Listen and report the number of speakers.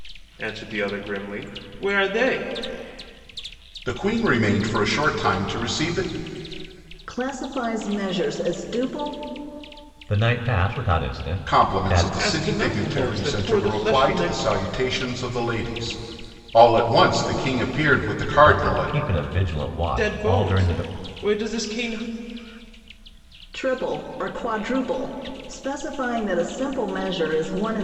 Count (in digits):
4